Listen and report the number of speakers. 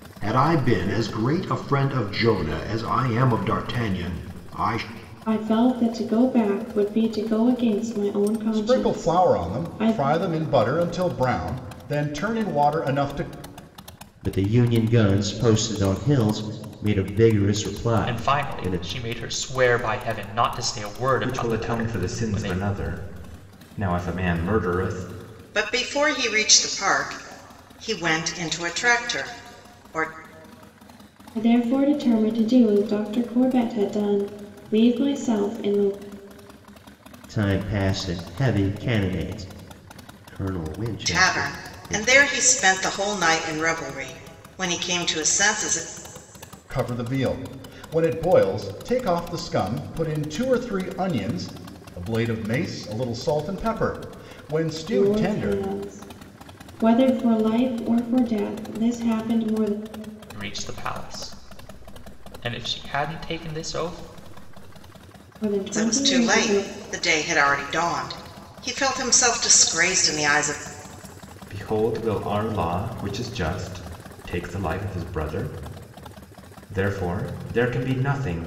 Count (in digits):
7